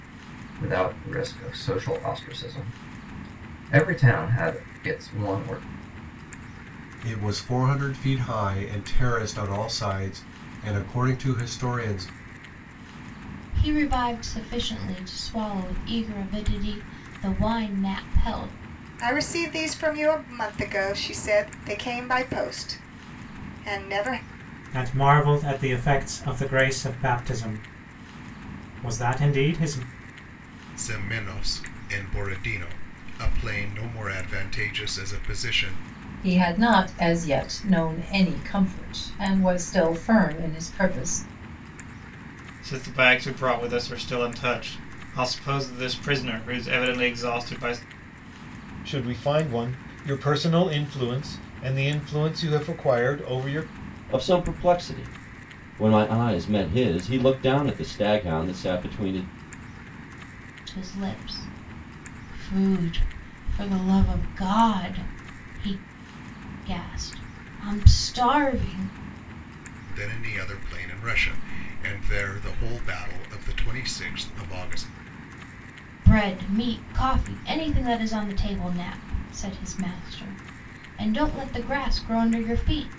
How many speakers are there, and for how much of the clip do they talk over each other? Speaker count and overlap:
10, no overlap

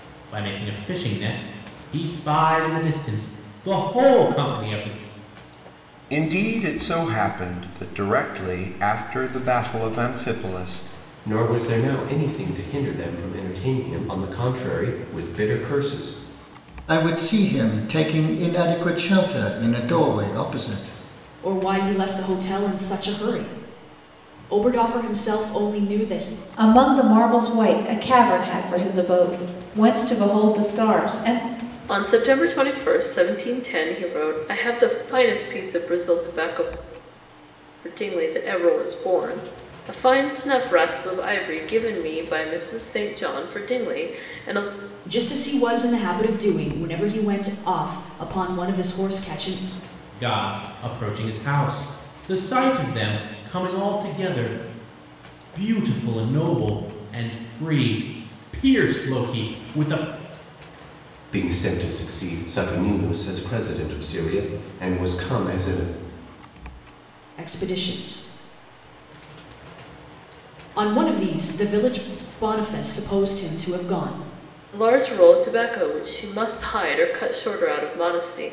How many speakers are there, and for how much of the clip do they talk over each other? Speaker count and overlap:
7, no overlap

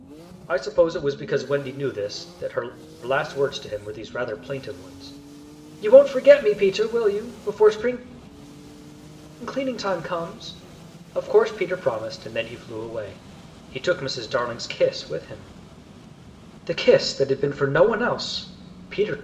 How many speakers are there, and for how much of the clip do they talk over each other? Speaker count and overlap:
1, no overlap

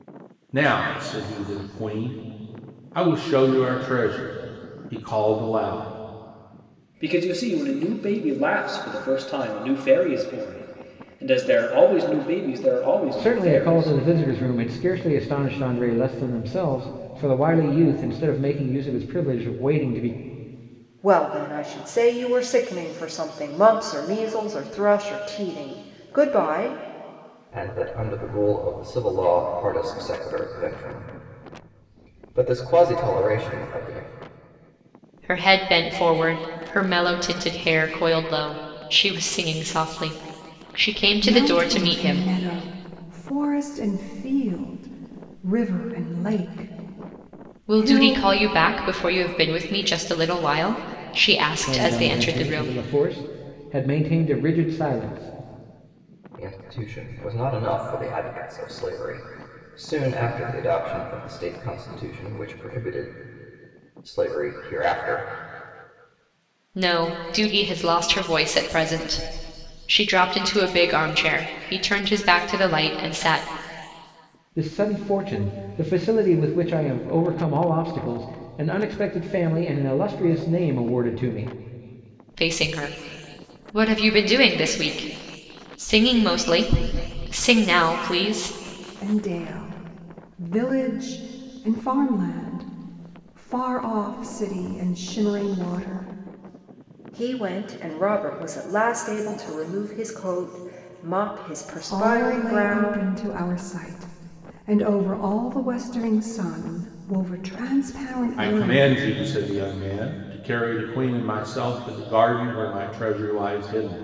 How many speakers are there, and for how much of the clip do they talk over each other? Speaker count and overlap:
7, about 5%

